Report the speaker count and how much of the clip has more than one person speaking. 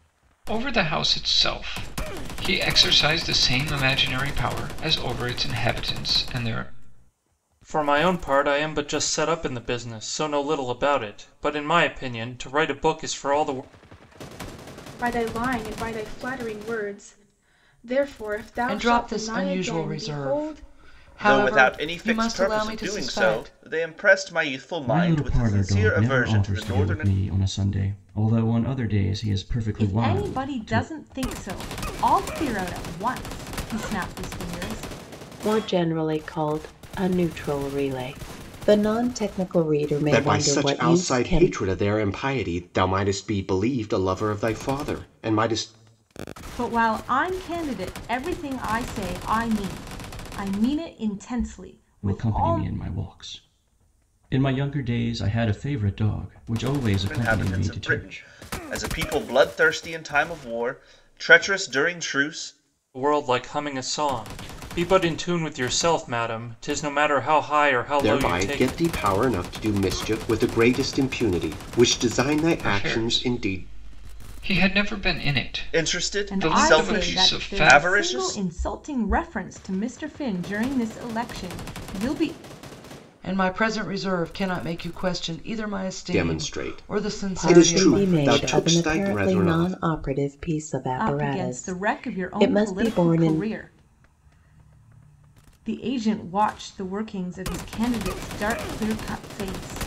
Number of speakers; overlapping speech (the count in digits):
9, about 22%